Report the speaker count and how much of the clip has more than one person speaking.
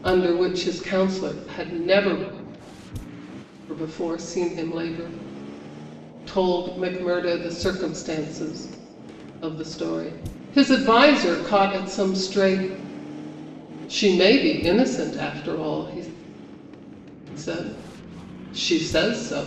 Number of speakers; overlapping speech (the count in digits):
1, no overlap